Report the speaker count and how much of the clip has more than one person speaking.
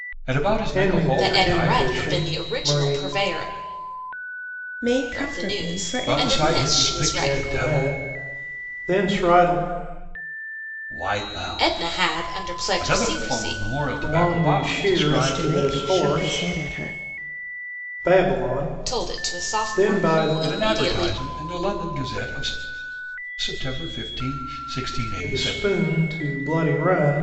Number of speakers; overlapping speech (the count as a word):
four, about 46%